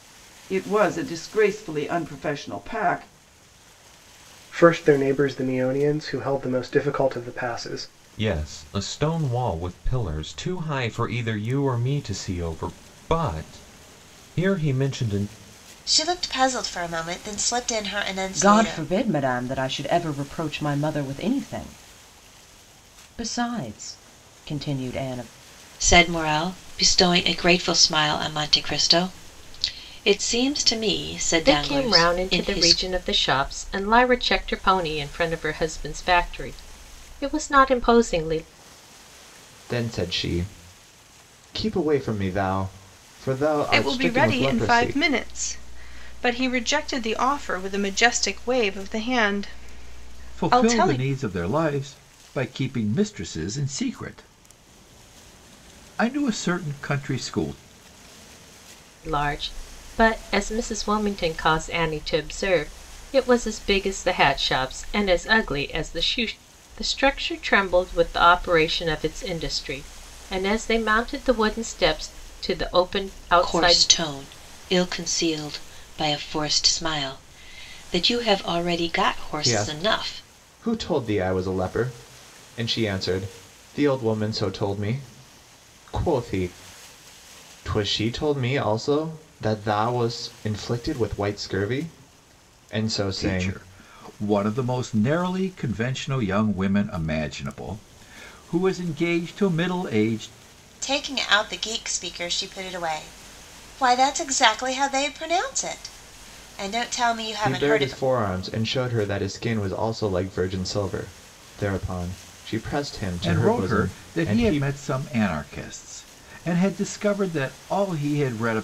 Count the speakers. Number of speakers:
10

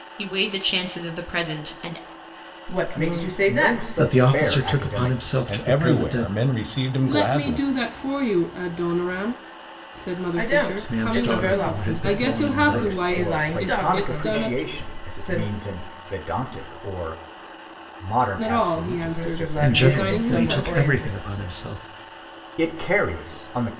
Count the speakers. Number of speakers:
6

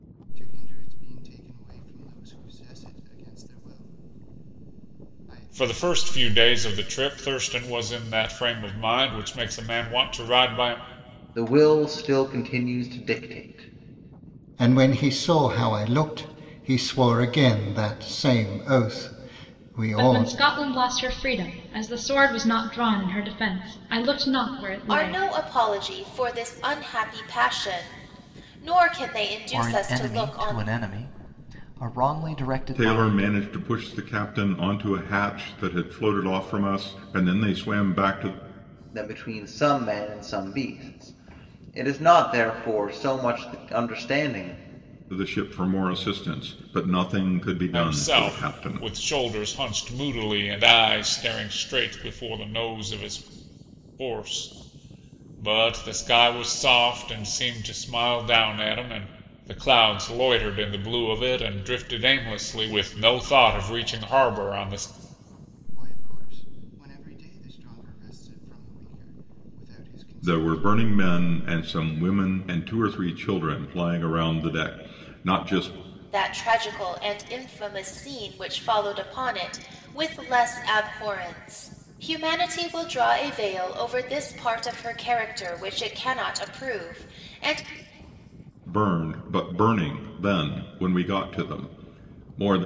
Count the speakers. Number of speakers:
8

